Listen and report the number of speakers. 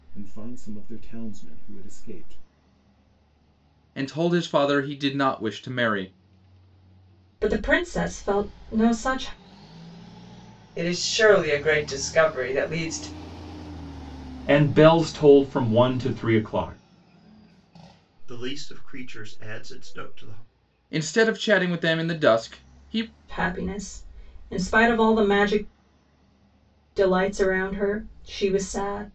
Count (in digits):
6